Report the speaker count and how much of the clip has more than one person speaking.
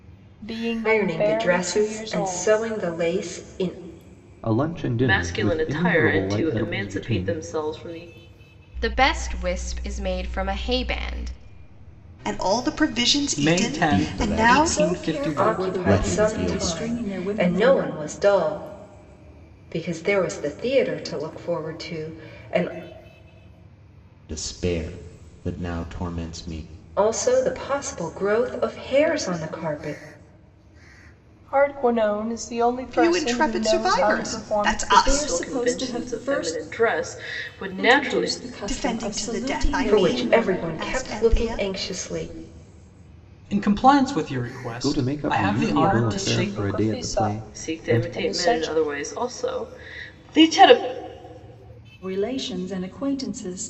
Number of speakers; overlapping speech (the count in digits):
9, about 37%